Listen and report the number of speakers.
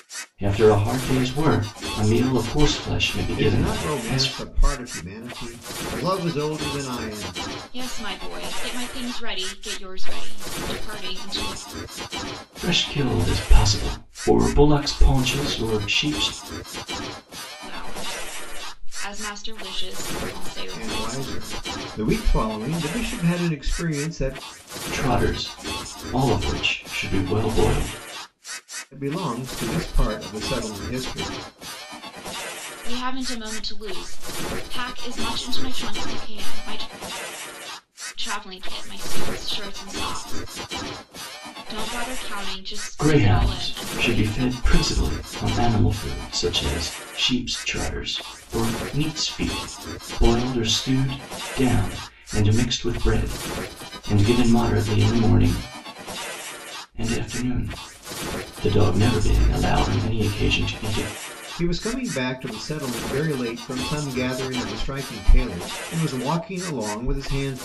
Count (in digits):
3